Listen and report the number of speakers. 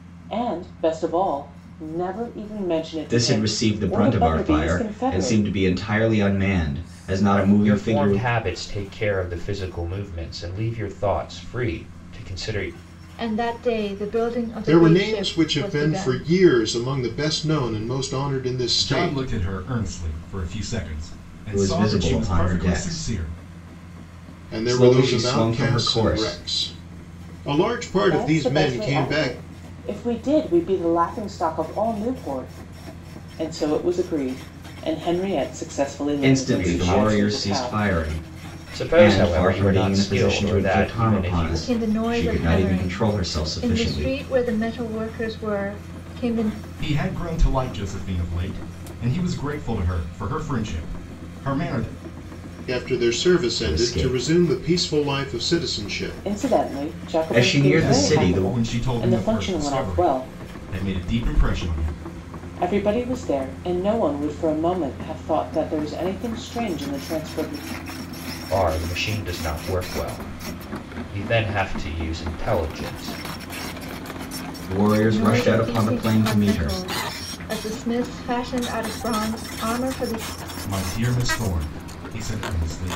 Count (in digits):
6